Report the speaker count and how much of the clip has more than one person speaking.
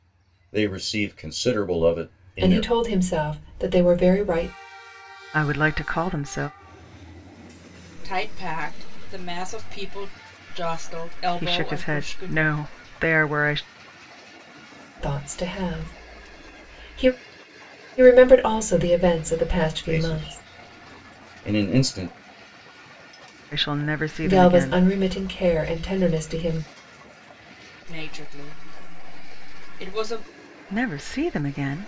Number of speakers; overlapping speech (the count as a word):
four, about 9%